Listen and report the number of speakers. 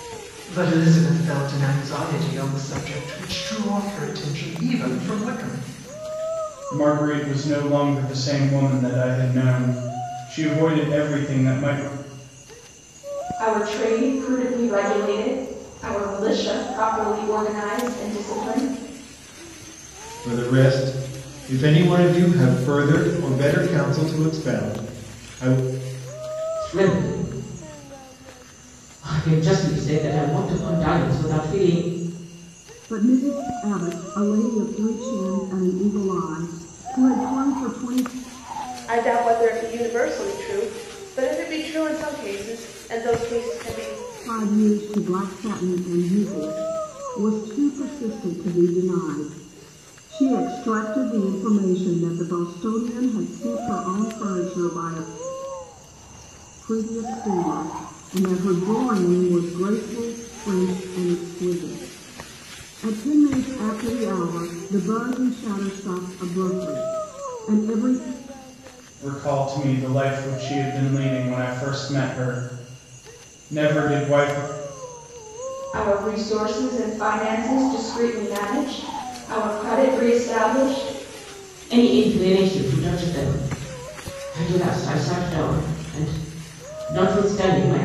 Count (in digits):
7